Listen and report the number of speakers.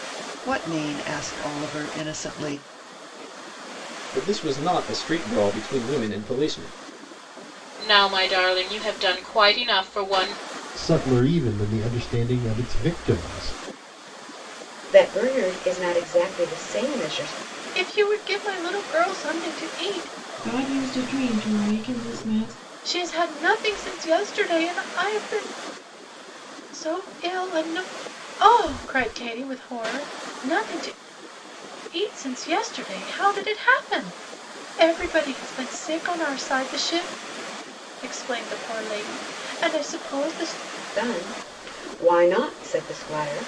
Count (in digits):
7